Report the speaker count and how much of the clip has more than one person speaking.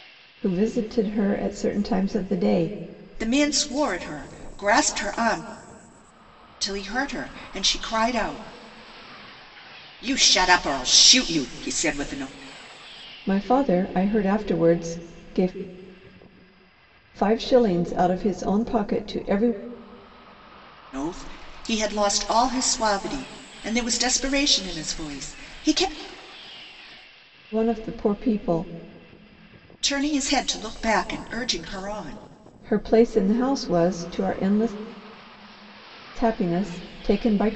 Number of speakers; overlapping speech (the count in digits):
2, no overlap